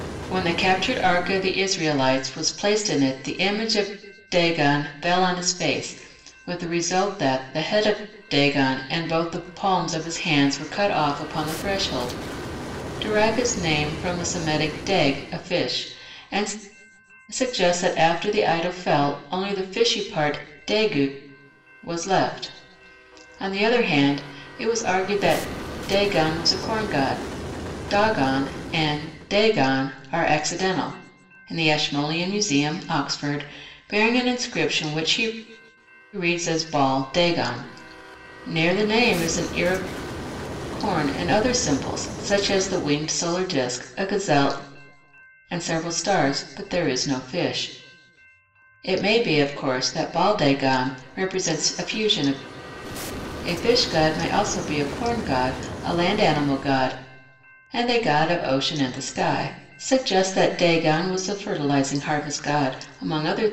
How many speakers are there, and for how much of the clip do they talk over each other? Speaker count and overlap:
1, no overlap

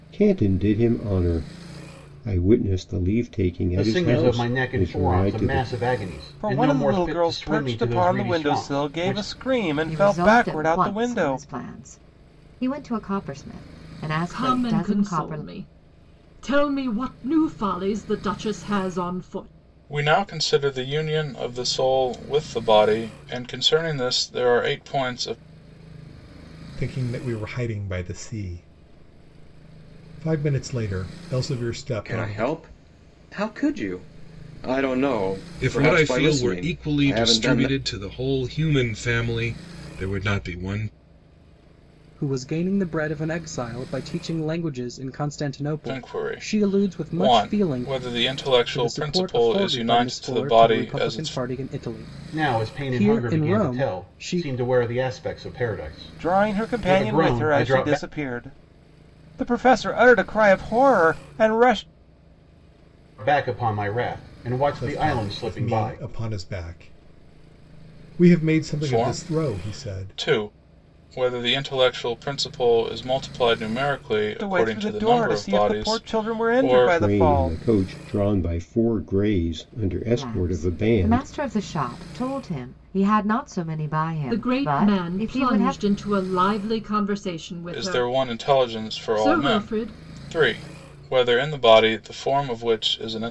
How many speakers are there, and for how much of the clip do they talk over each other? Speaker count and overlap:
10, about 33%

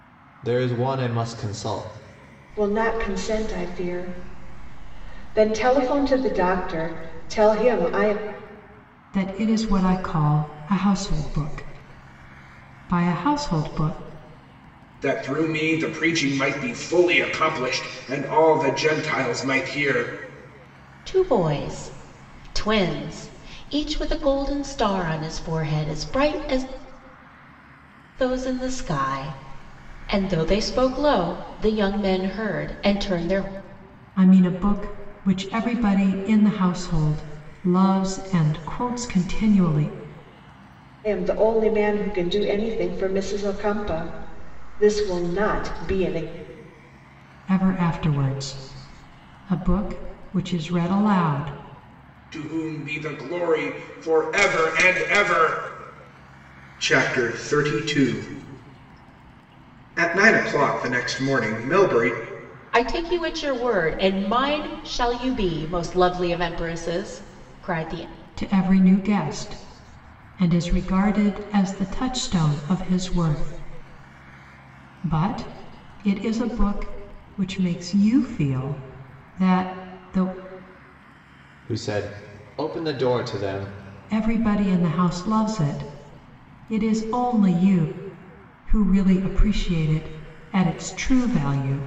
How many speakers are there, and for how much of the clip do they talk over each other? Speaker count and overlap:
5, no overlap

